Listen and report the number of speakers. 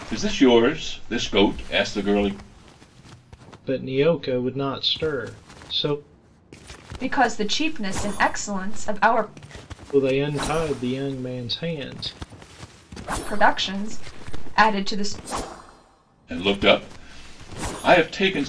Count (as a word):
three